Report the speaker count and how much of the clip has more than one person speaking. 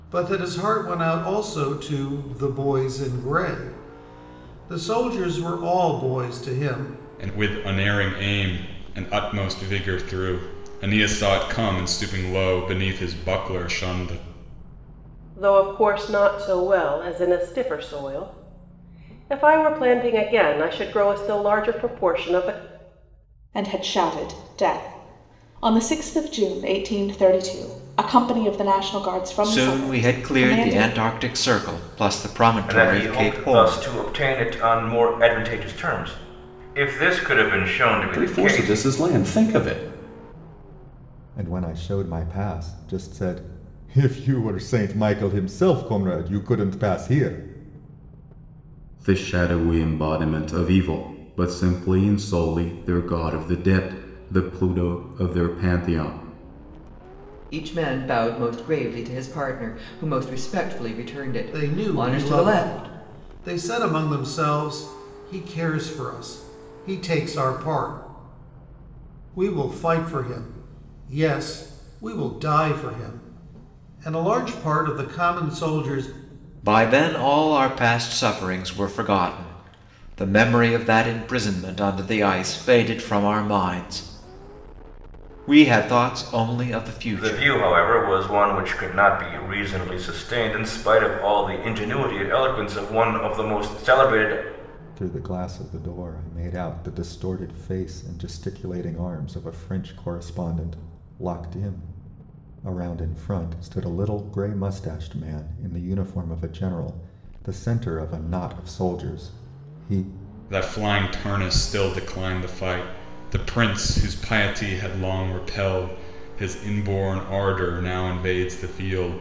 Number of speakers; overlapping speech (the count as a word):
ten, about 5%